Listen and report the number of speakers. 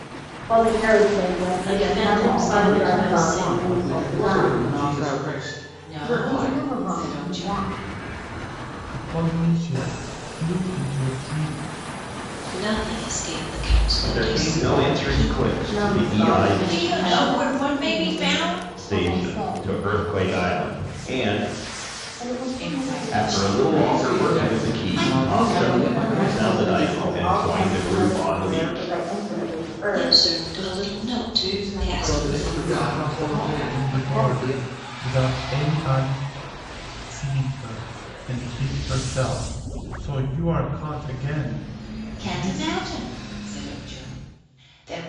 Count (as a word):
ten